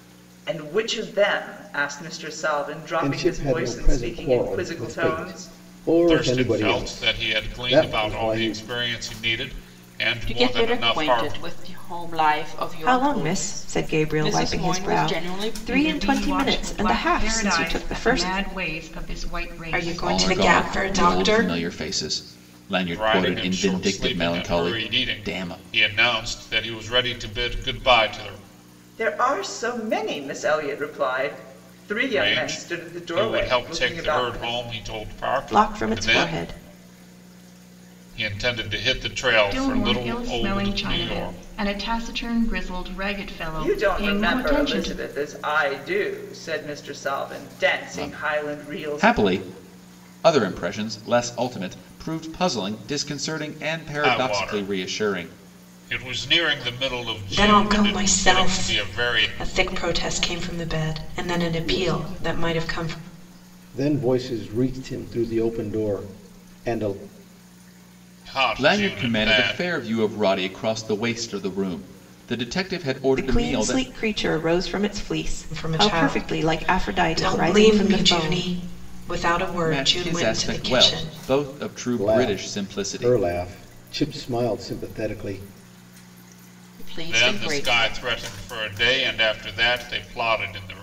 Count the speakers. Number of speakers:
8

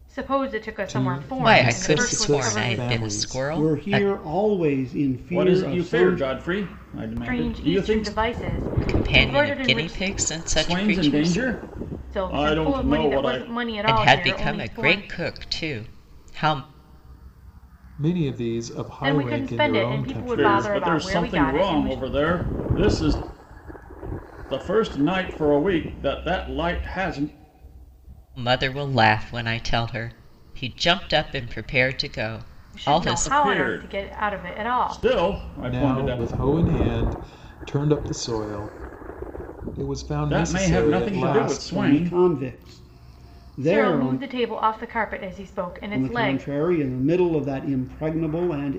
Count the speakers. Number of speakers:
5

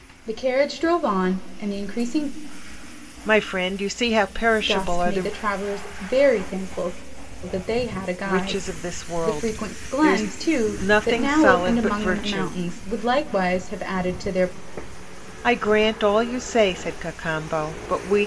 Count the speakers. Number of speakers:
2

